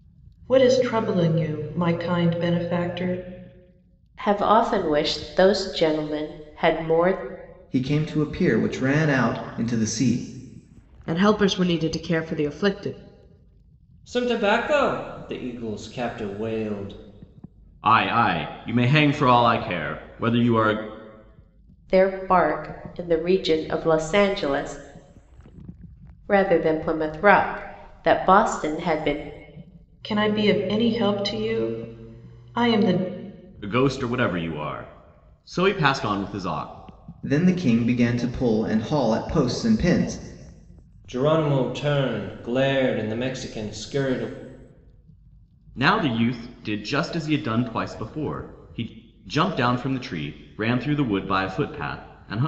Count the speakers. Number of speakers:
6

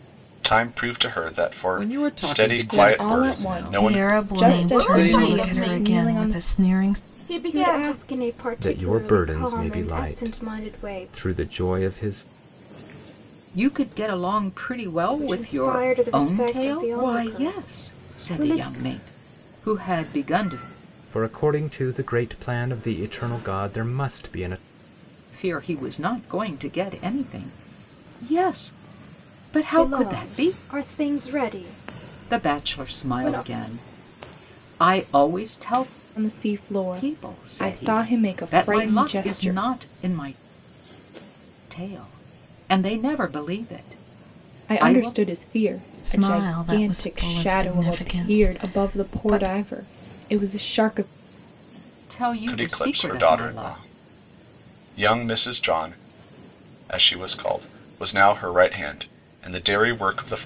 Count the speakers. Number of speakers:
8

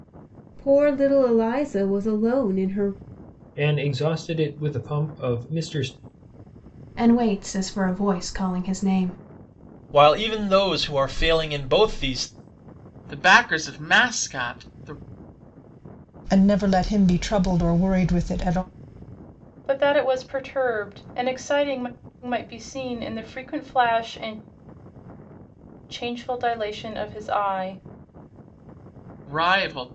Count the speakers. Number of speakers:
7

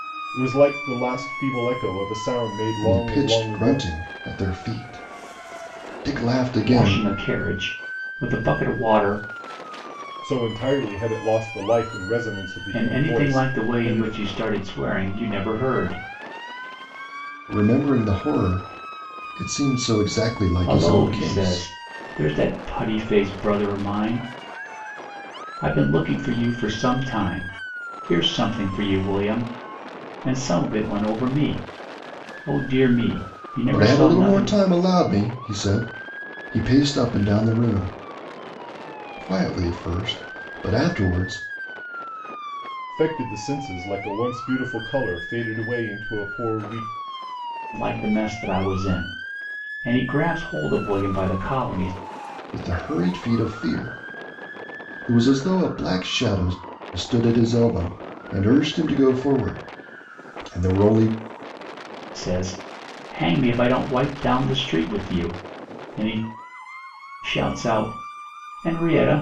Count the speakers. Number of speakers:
3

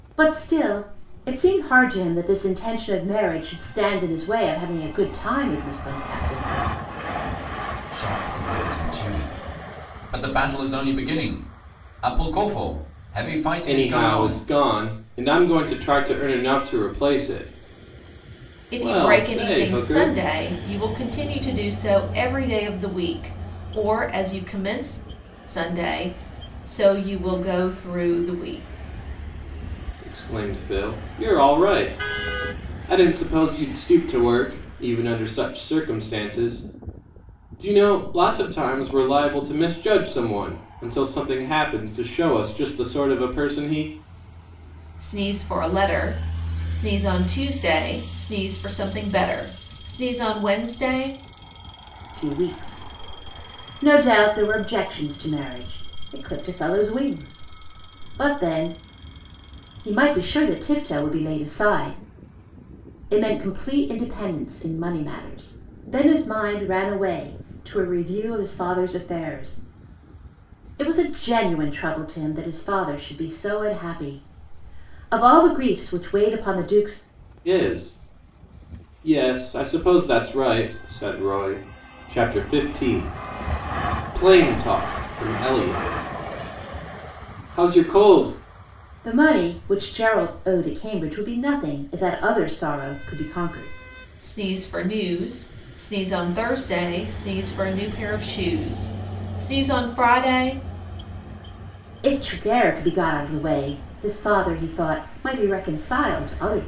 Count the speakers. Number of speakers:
4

